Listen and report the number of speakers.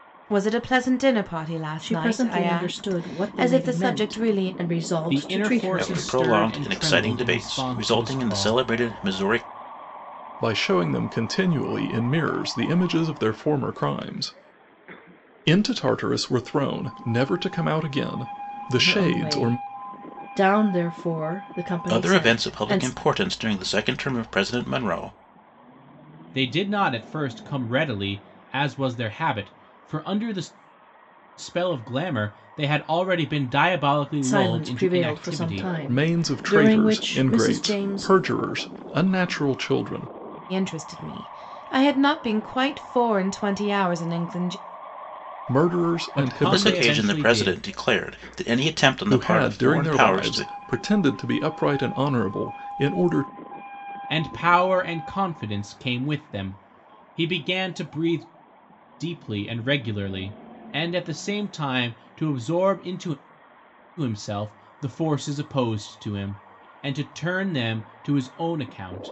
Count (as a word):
five